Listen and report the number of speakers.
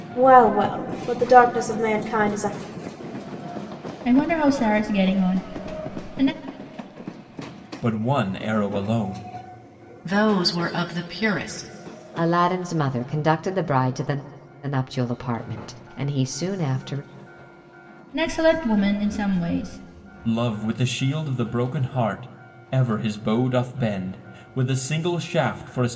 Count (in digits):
5